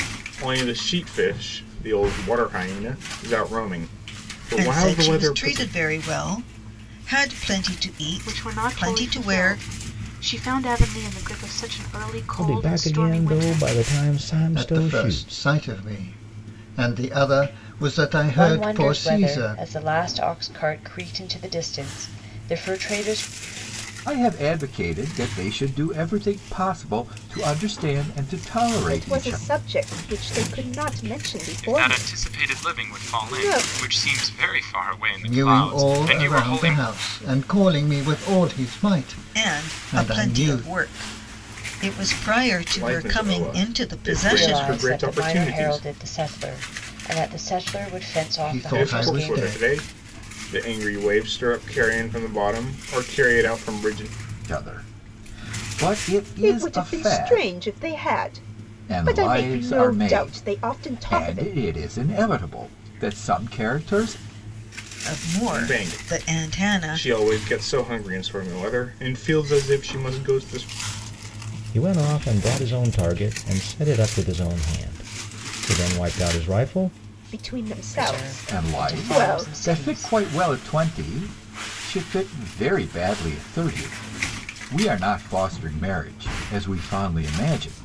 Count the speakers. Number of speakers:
nine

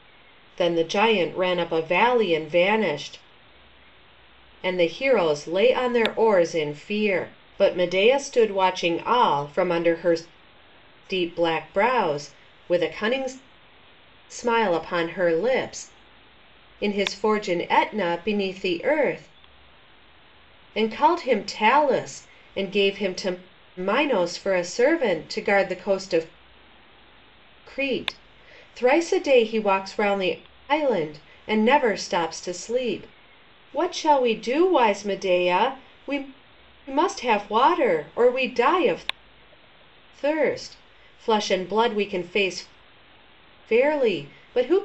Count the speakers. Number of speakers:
one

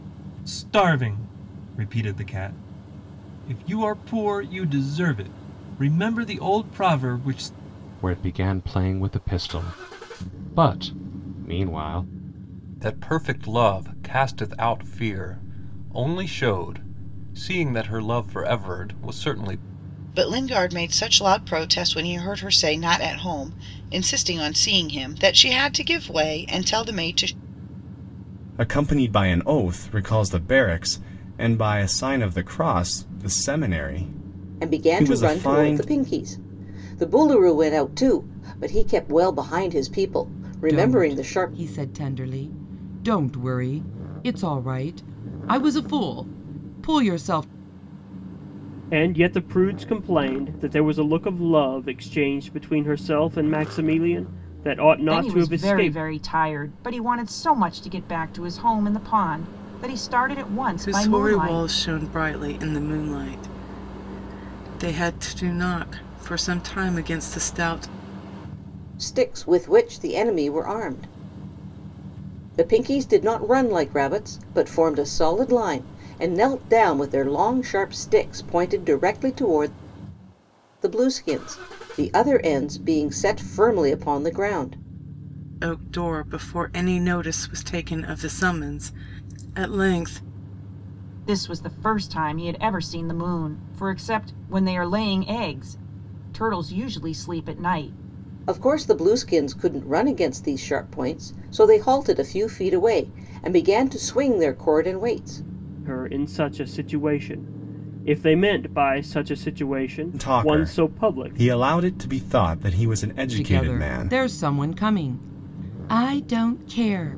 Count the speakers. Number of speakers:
ten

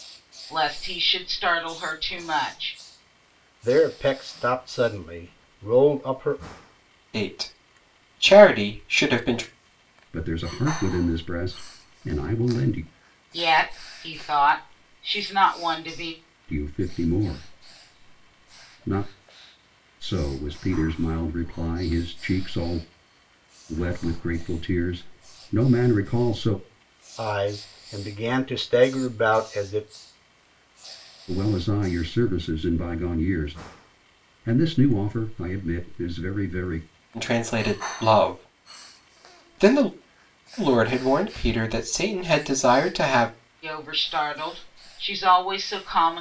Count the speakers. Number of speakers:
four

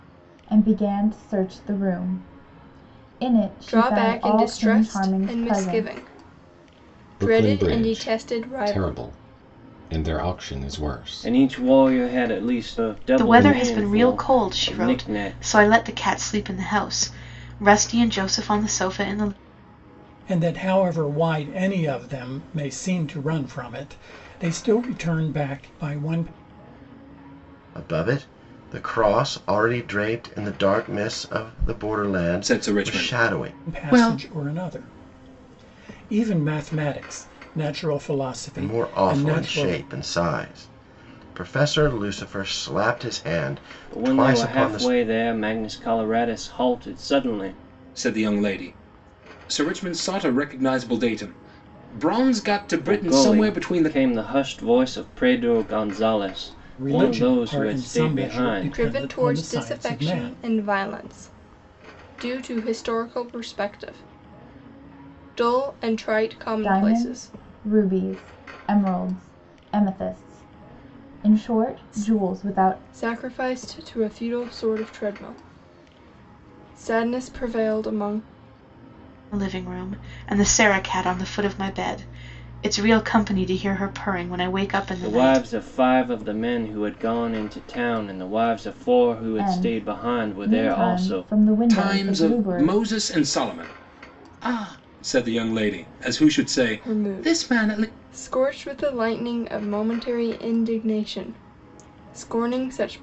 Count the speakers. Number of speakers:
eight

